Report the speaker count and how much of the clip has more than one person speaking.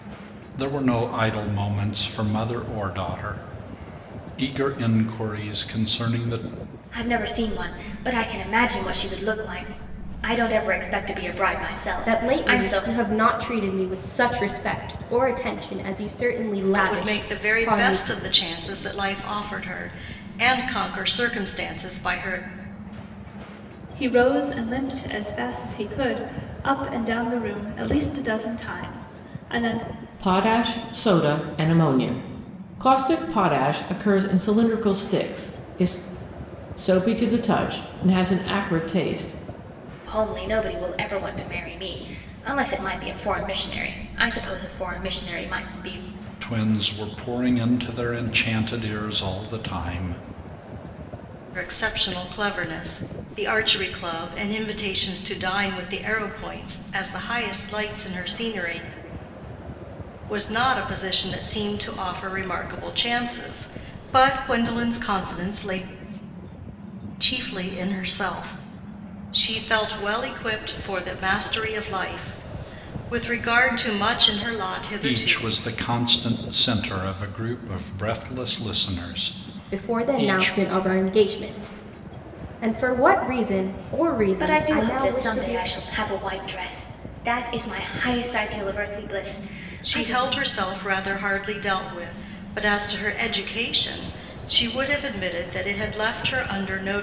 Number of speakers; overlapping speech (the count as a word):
six, about 6%